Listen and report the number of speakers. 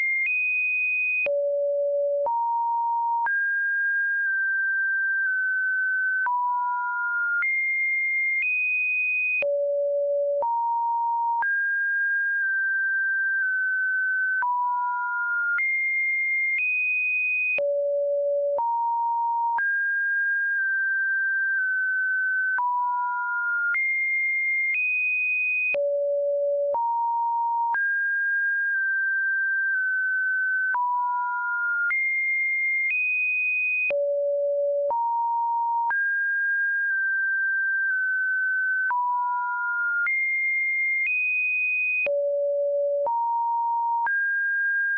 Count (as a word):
zero